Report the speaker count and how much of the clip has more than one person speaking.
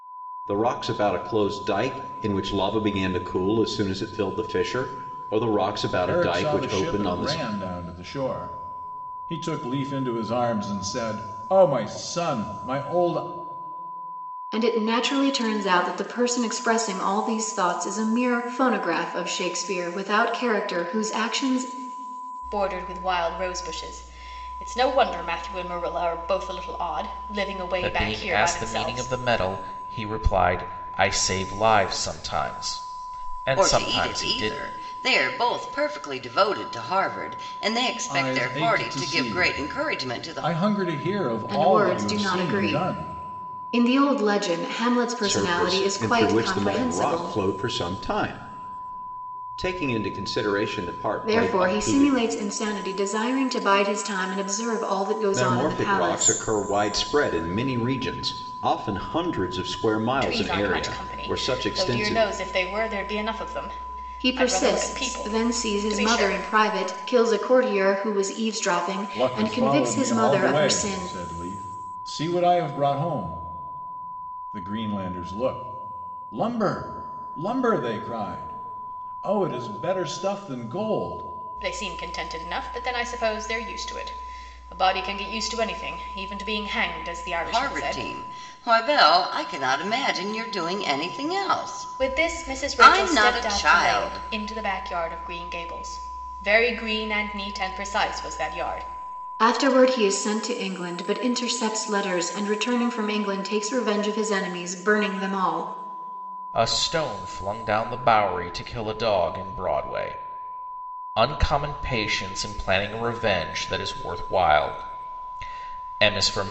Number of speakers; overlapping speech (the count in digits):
6, about 19%